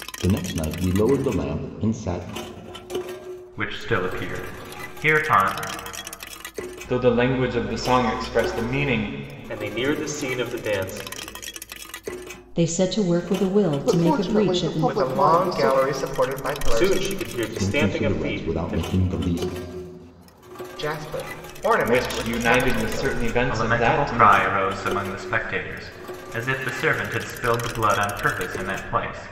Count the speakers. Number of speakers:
7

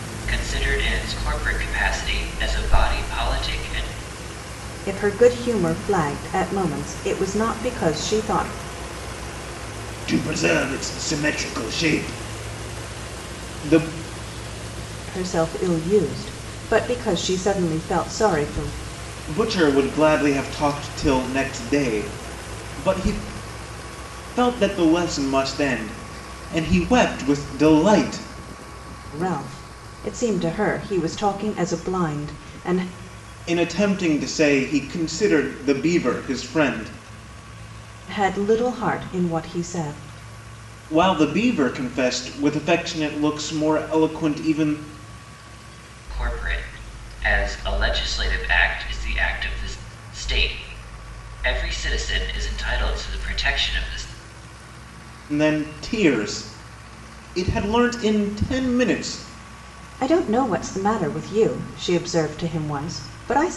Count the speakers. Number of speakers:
3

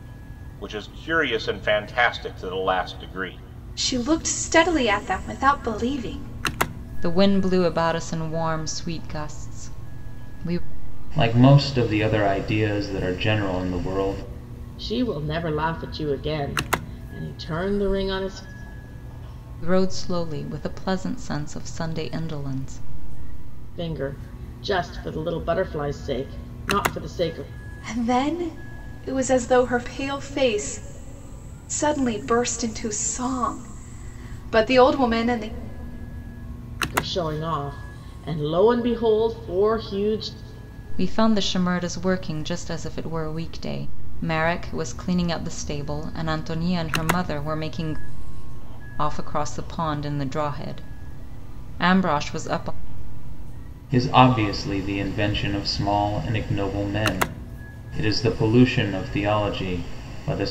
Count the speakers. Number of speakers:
5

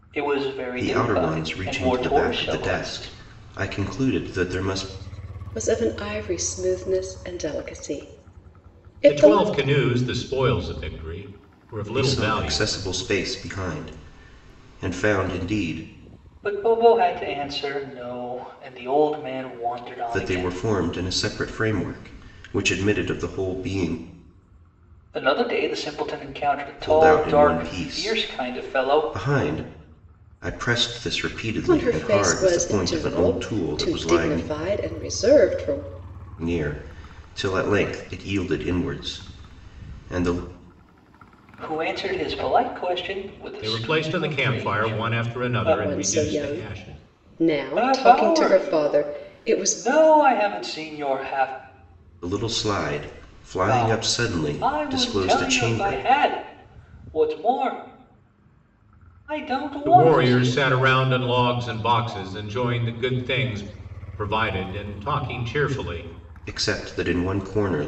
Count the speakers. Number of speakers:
4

